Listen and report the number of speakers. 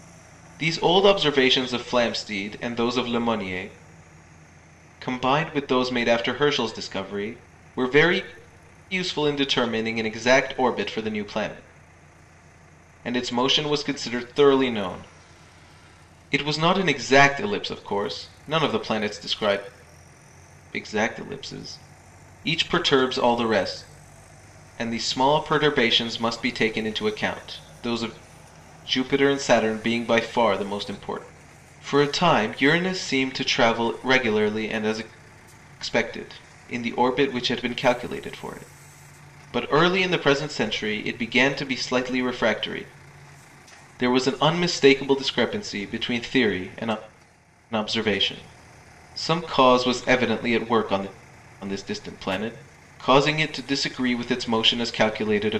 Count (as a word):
one